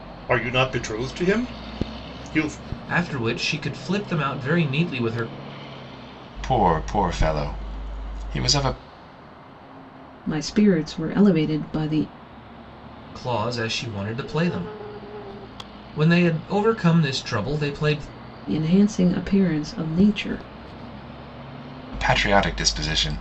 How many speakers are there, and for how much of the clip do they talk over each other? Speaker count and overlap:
4, no overlap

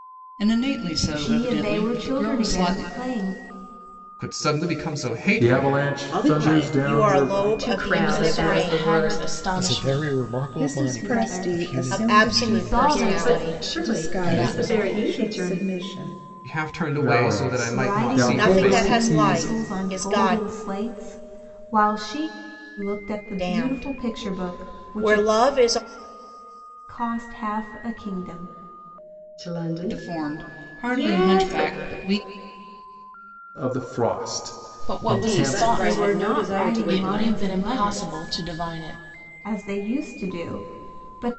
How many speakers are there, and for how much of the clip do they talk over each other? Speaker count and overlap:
10, about 54%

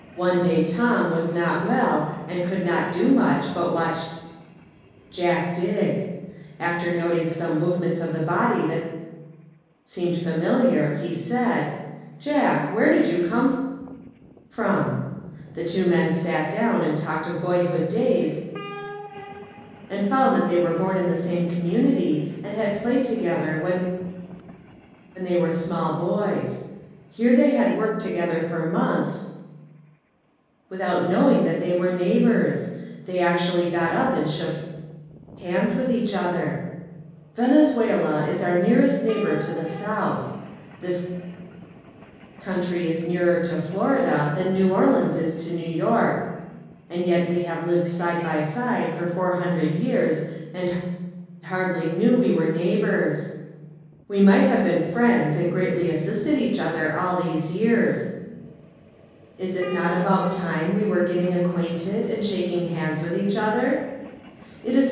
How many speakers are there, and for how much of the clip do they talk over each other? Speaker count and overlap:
1, no overlap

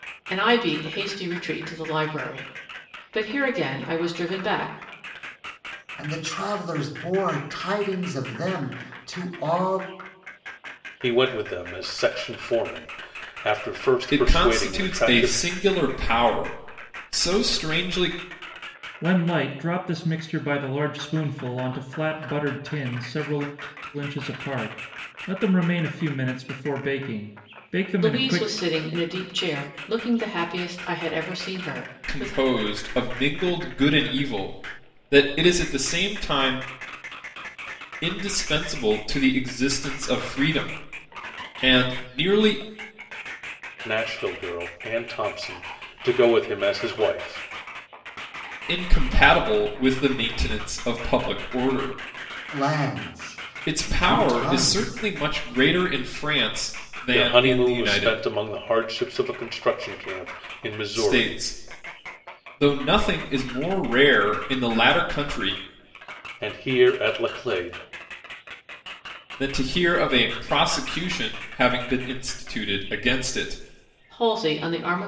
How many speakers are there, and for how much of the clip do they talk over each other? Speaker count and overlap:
5, about 7%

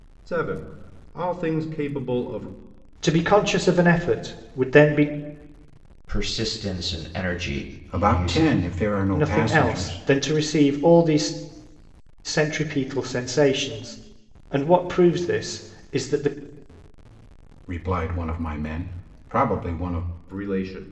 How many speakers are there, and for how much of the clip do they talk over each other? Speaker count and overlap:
4, about 7%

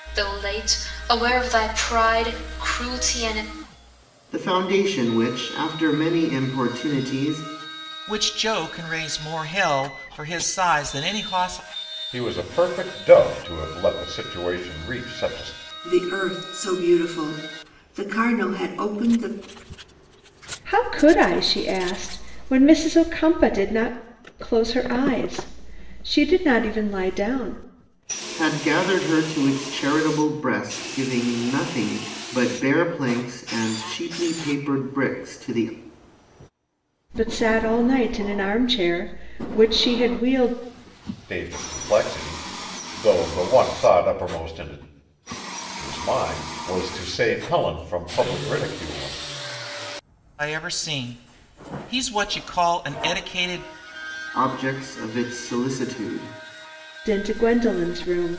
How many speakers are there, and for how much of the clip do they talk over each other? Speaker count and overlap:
6, no overlap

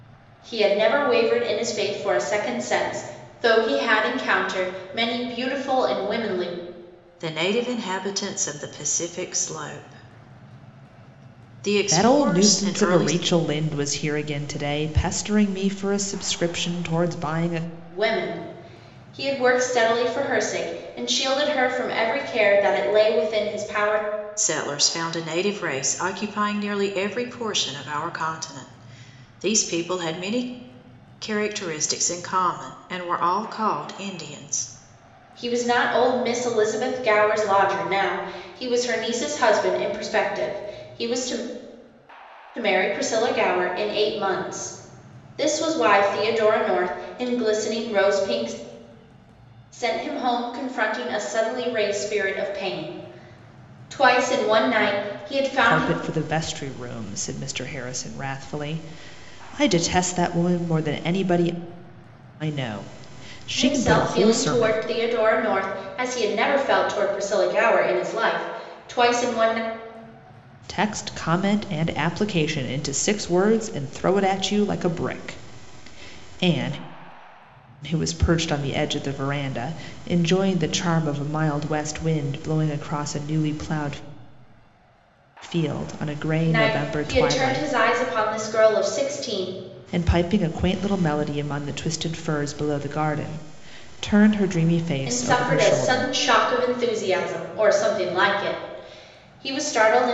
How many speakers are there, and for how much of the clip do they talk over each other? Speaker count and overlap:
3, about 5%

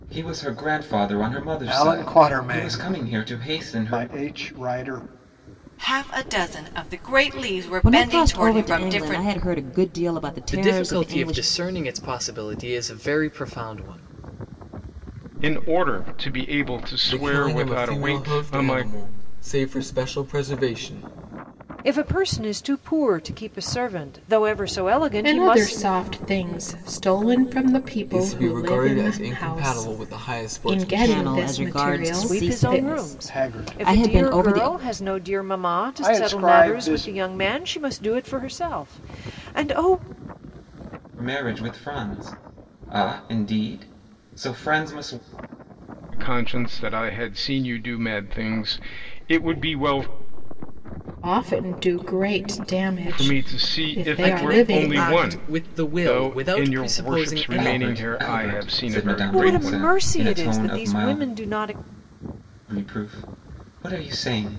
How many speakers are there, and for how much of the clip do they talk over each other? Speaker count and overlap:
9, about 38%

